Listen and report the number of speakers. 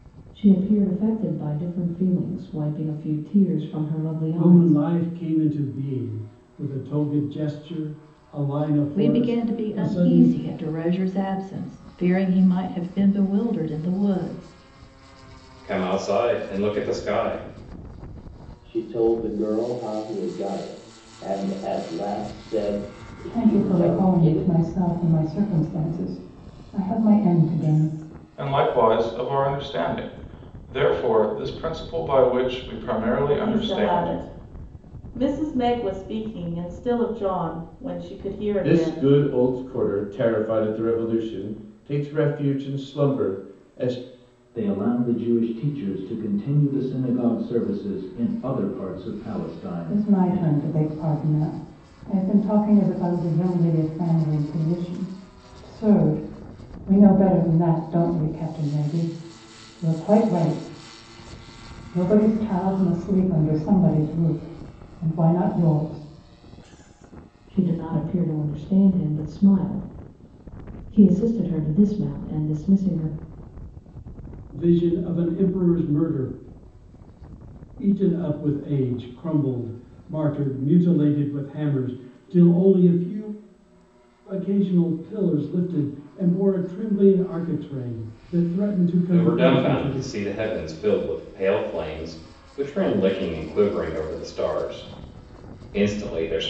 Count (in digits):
10